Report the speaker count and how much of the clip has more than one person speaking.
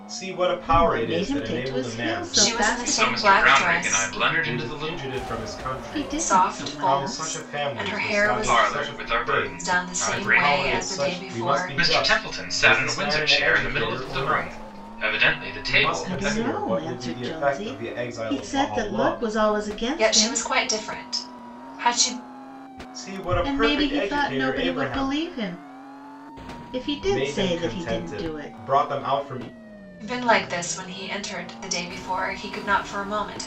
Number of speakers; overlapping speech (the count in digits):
4, about 61%